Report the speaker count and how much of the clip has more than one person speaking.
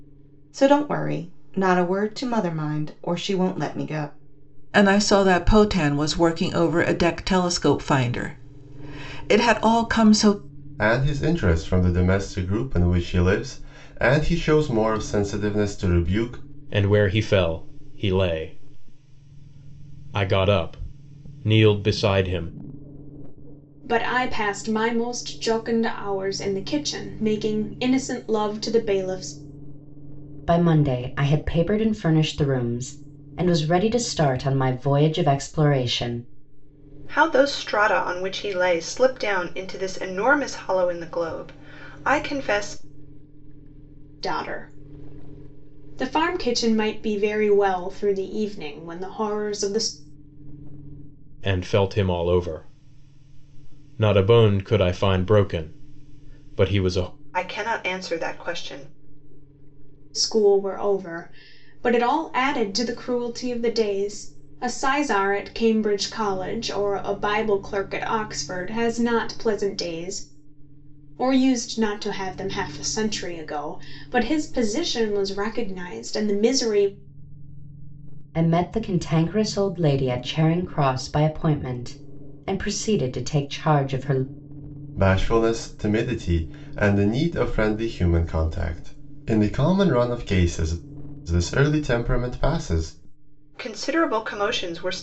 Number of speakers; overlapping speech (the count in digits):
7, no overlap